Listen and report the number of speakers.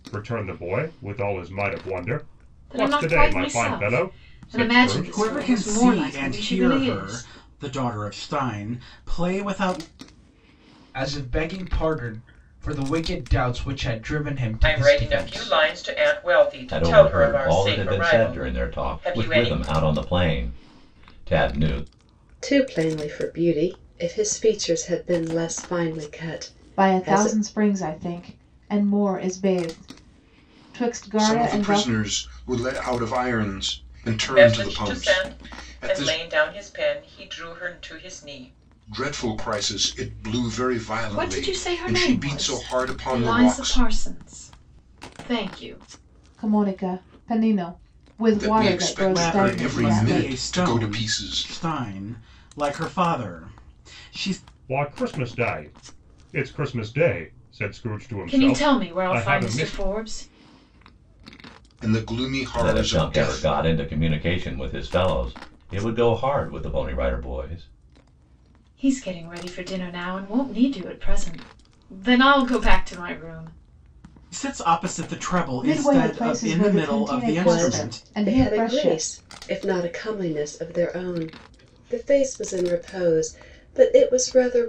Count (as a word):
nine